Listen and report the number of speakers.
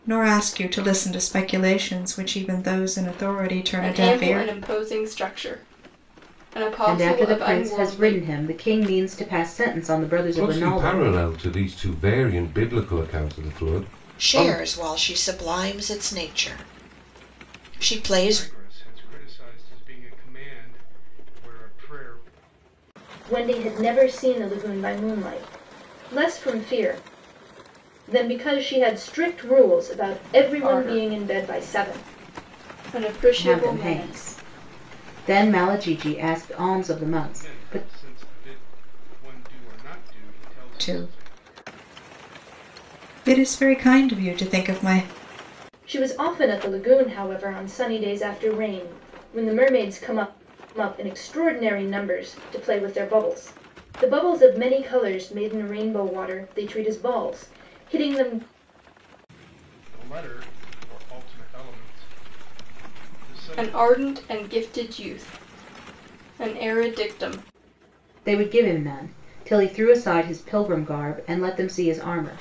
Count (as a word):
seven